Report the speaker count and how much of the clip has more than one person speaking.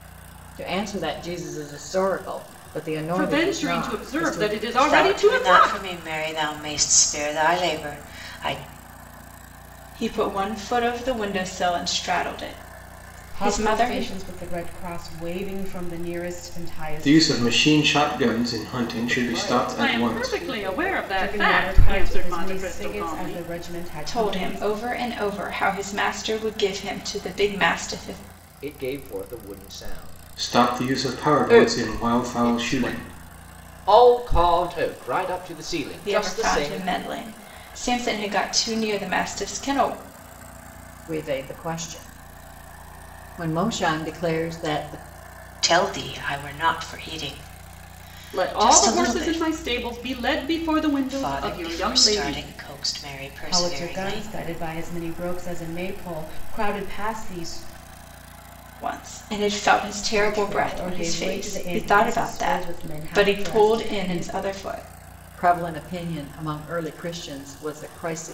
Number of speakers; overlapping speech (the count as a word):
seven, about 30%